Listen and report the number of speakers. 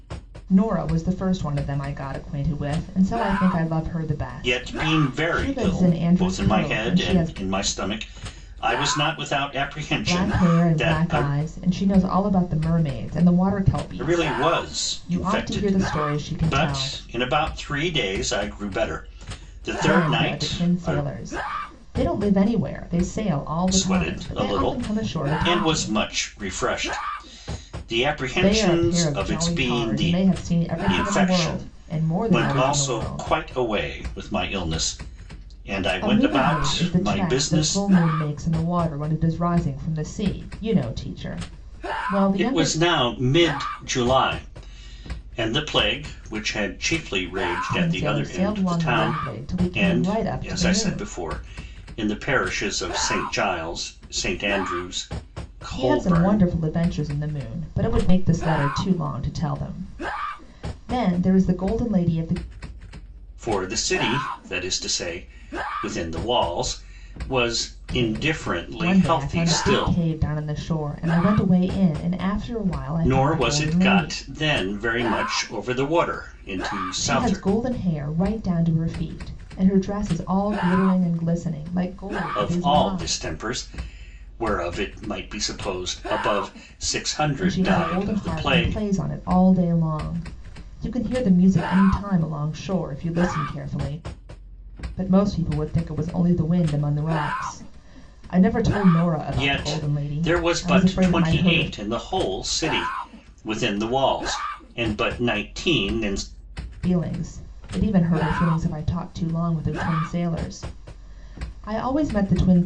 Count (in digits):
2